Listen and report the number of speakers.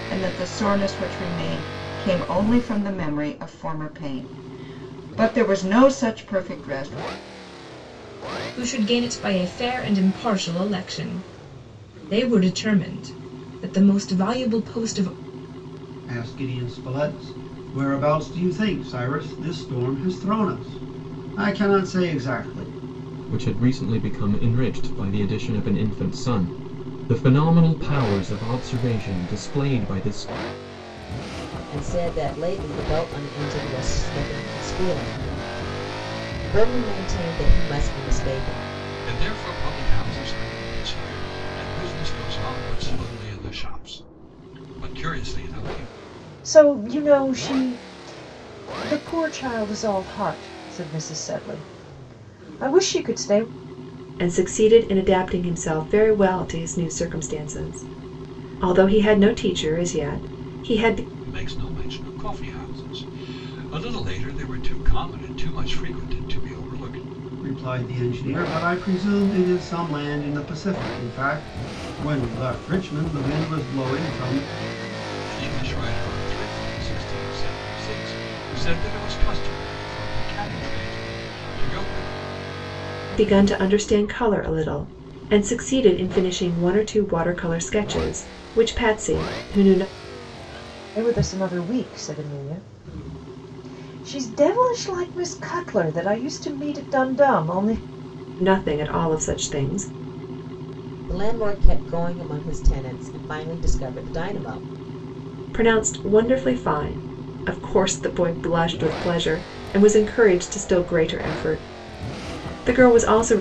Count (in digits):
8